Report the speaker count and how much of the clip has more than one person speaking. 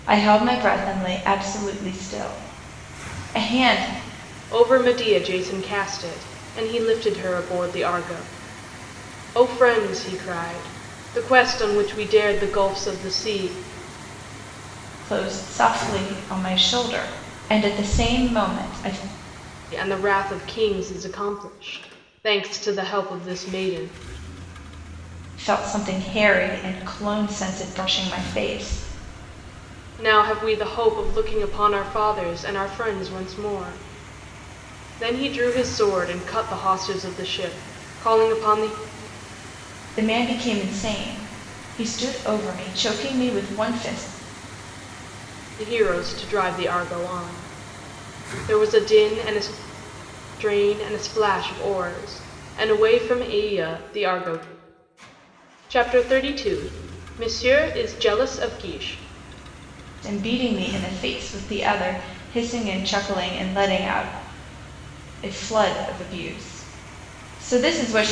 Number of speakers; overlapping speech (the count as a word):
two, no overlap